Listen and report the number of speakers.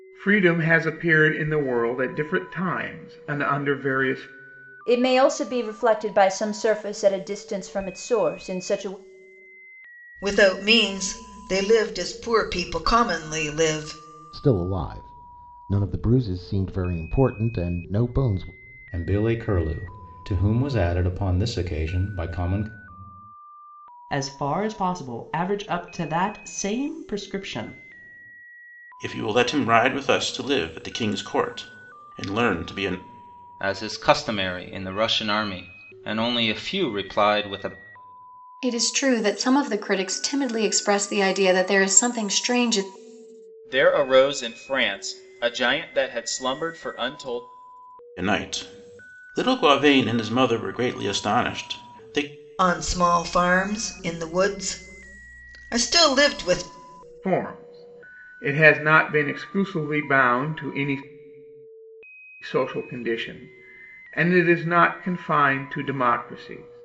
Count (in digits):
10